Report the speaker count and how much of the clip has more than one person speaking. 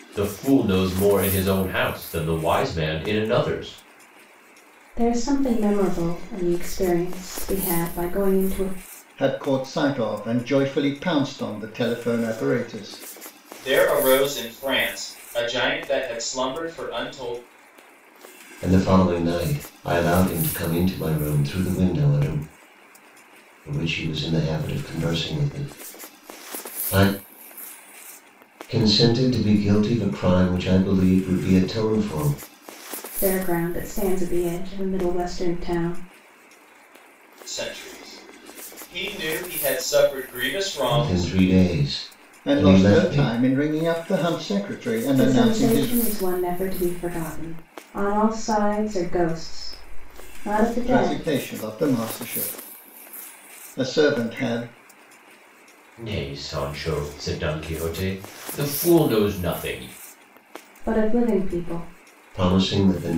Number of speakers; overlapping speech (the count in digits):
5, about 4%